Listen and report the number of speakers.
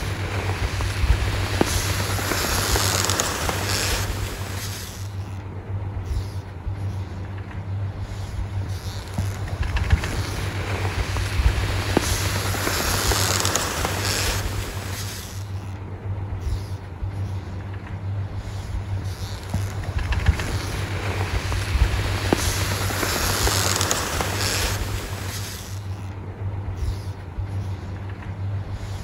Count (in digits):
0